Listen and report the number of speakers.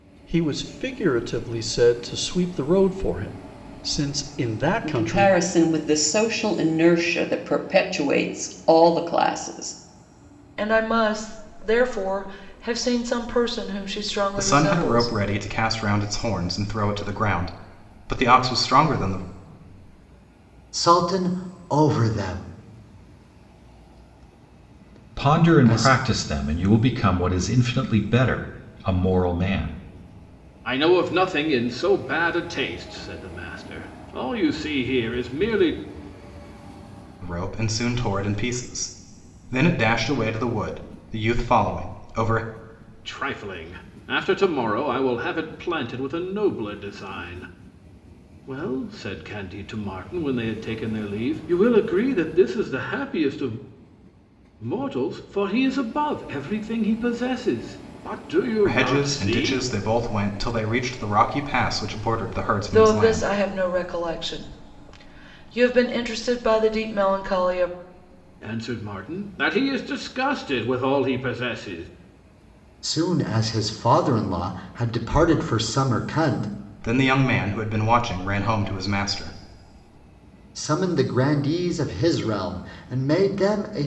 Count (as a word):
seven